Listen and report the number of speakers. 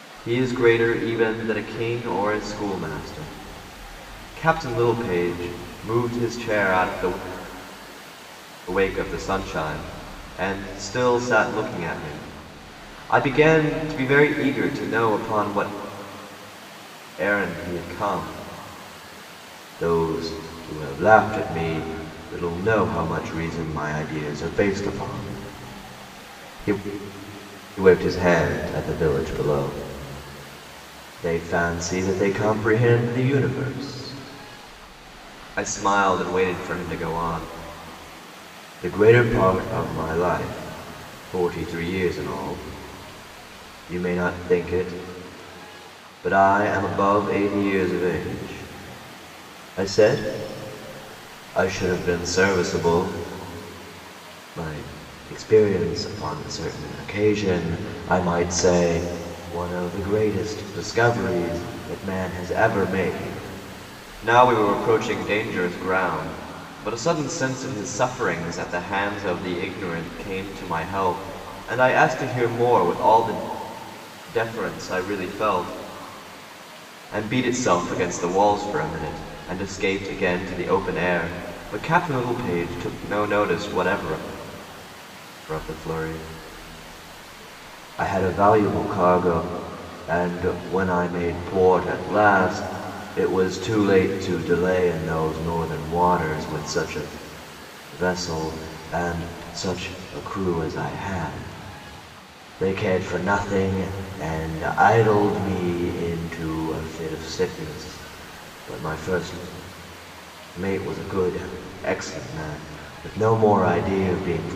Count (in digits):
1